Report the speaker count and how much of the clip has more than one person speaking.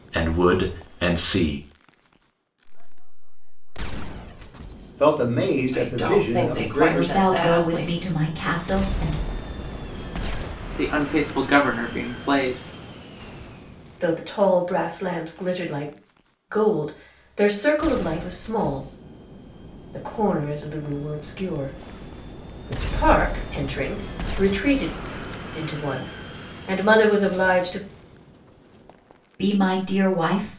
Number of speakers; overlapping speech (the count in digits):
7, about 7%